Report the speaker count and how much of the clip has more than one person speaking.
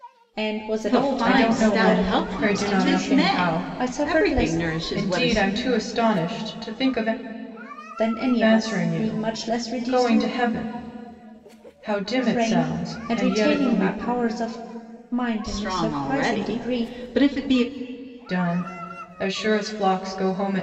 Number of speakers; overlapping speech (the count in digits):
3, about 46%